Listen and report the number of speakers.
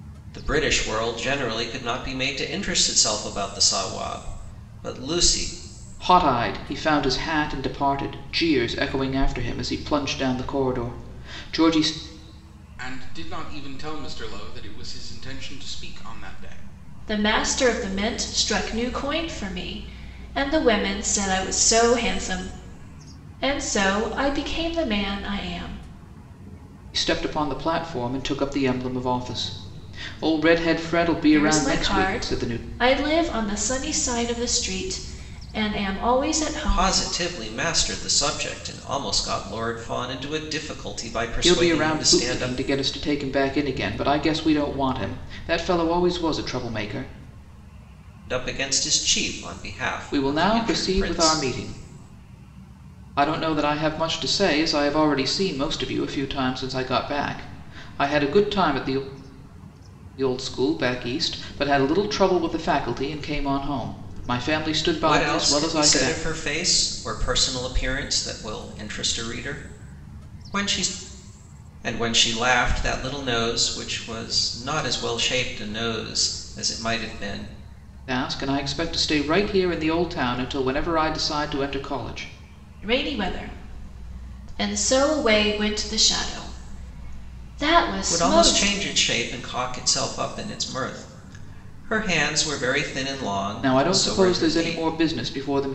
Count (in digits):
4